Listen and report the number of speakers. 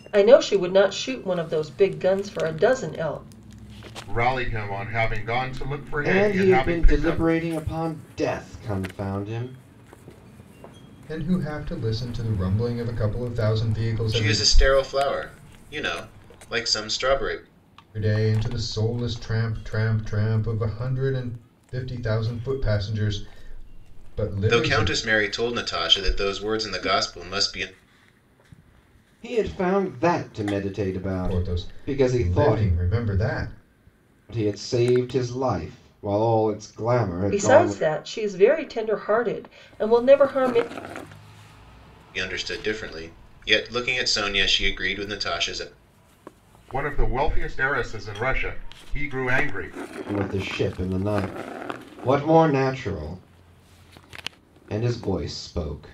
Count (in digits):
5